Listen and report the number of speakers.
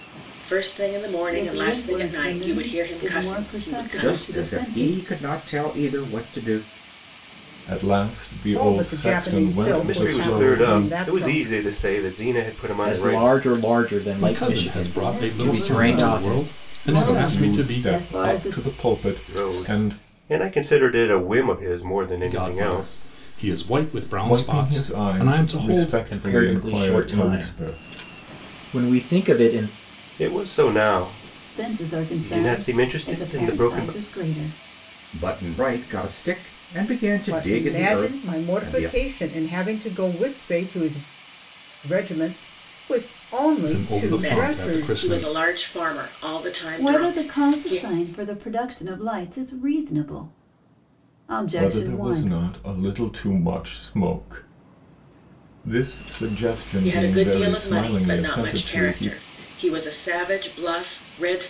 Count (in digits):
8